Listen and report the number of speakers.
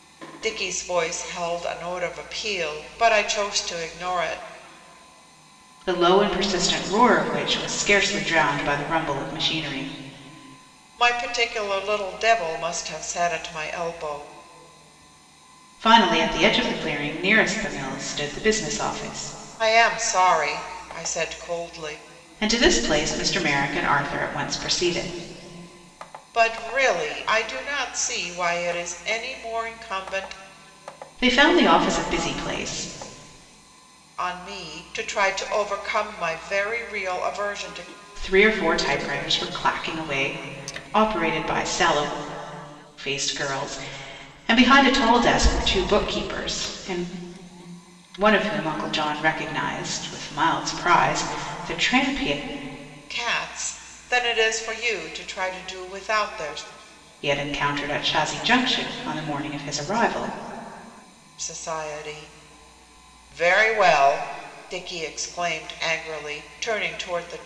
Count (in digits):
2